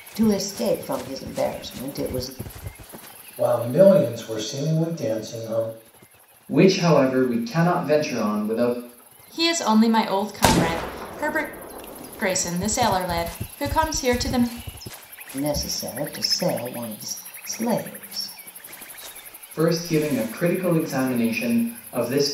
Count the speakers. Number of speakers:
four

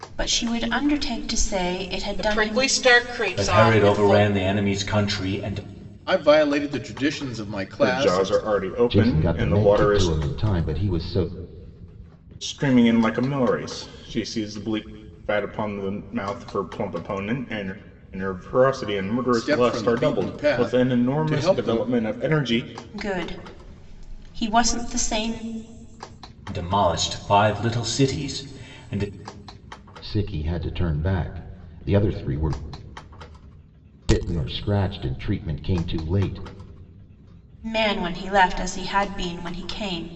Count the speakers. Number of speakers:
six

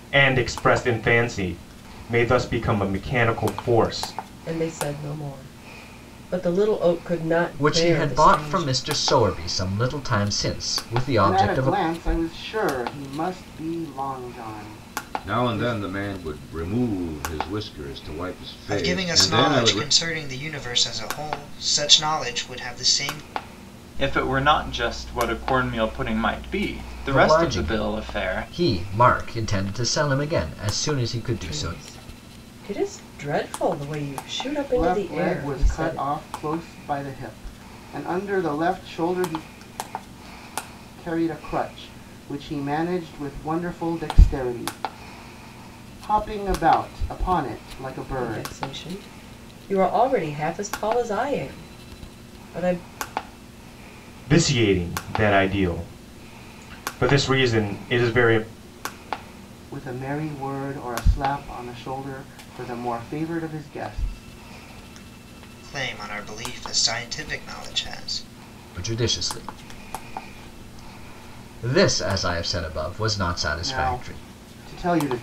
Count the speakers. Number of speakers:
seven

